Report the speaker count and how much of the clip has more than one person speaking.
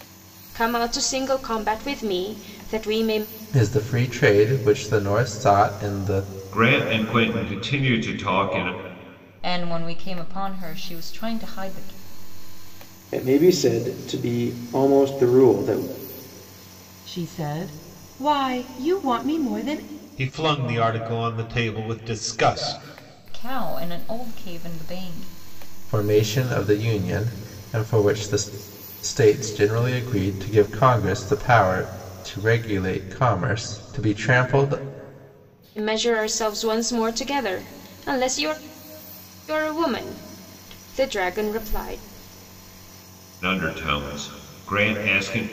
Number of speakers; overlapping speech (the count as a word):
seven, no overlap